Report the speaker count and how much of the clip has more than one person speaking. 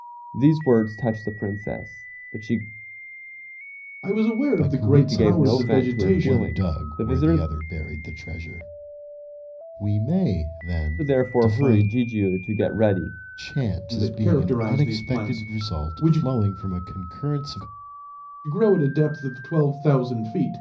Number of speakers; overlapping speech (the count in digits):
3, about 30%